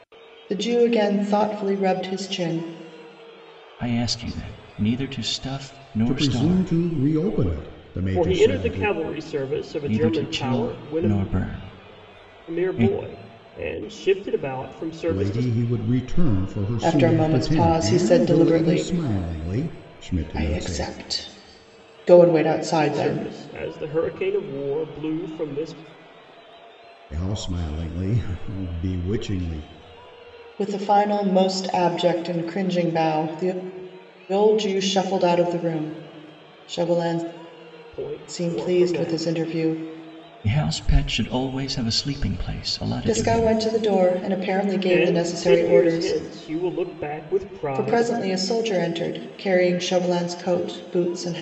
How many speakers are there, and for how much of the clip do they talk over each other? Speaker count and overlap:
four, about 20%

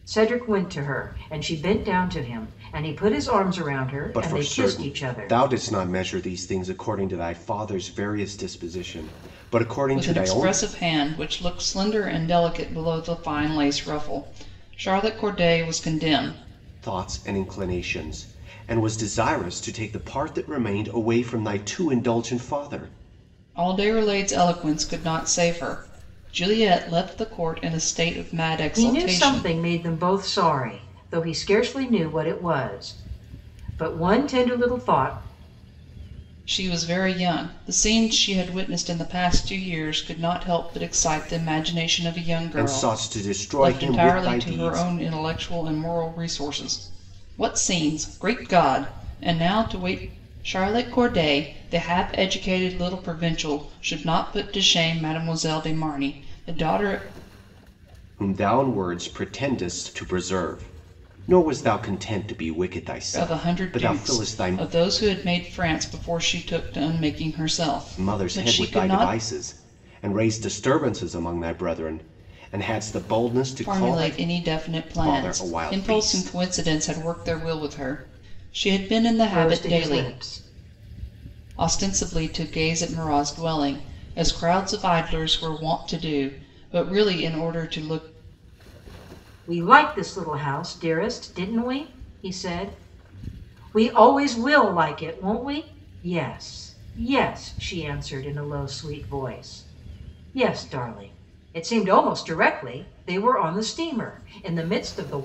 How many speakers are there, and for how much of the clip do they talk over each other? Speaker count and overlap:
three, about 9%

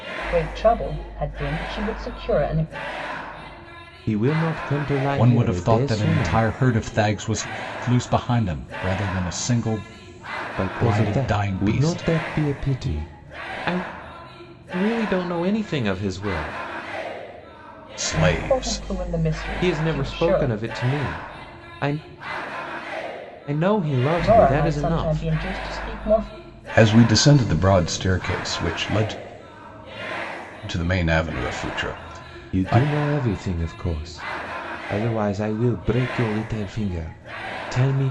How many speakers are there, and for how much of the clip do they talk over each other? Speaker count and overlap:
three, about 16%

